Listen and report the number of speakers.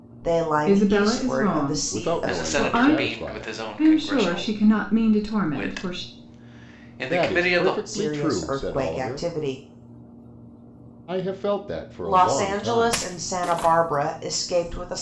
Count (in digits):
4